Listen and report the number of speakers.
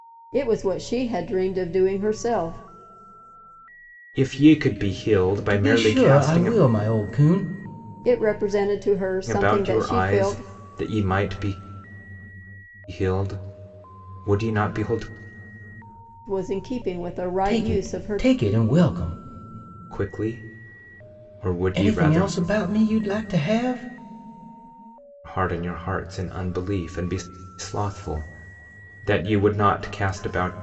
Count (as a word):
three